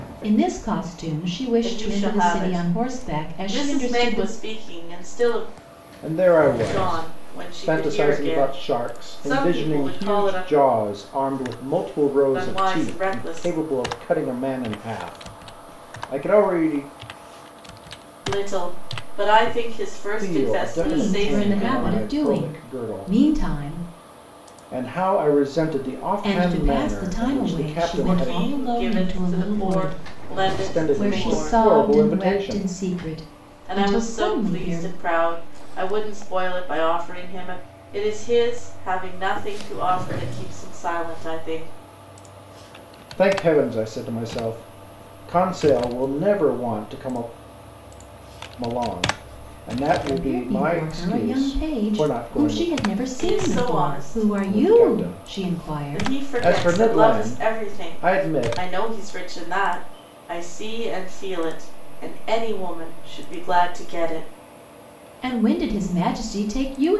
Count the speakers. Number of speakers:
three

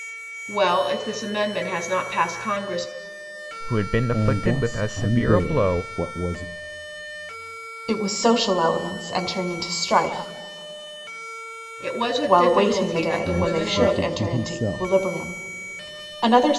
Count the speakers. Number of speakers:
four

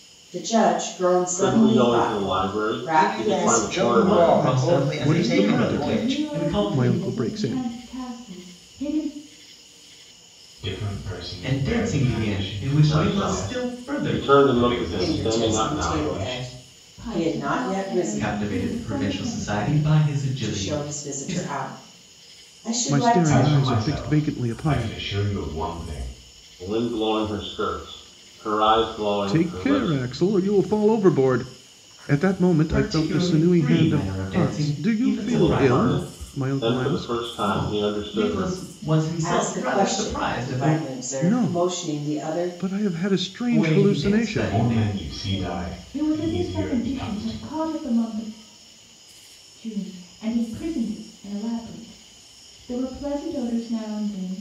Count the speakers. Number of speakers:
seven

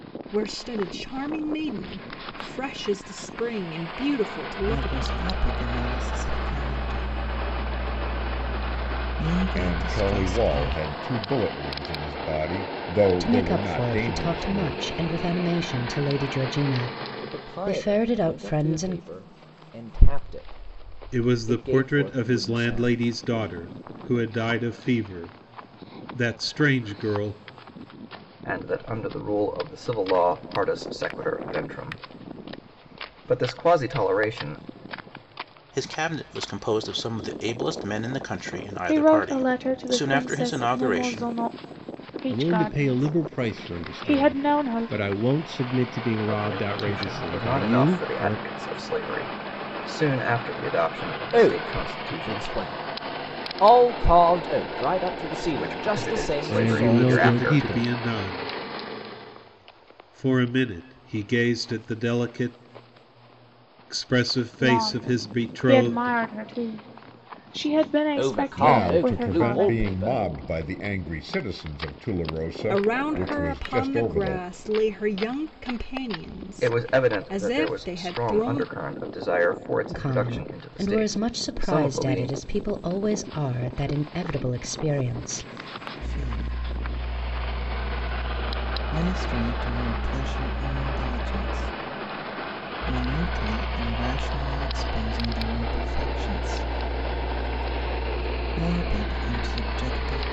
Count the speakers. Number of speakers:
ten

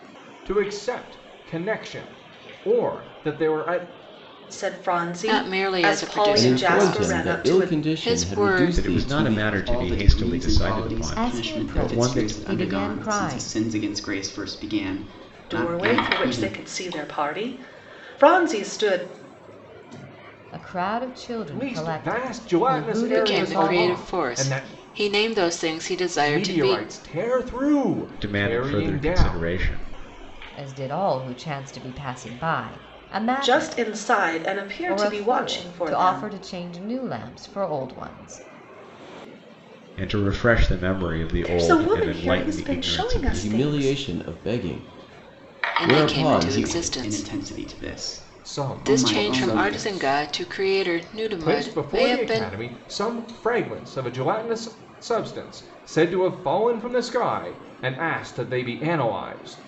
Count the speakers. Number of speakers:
seven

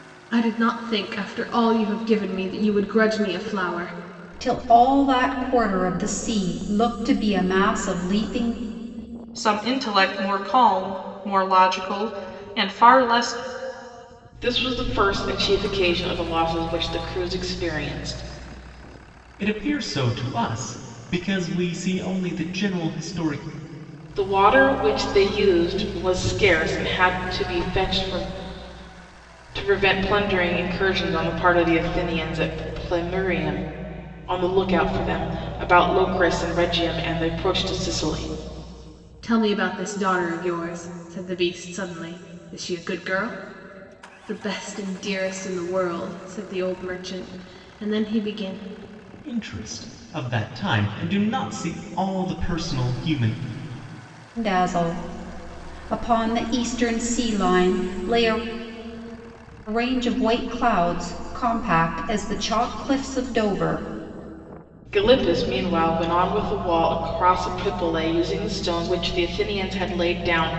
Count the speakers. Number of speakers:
five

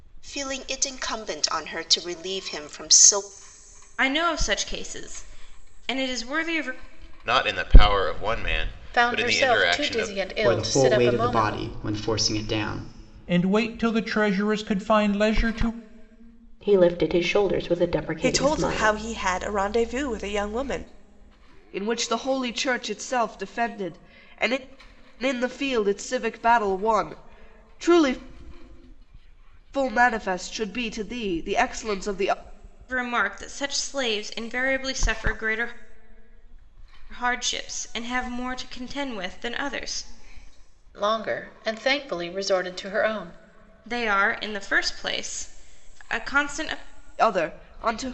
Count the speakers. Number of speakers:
nine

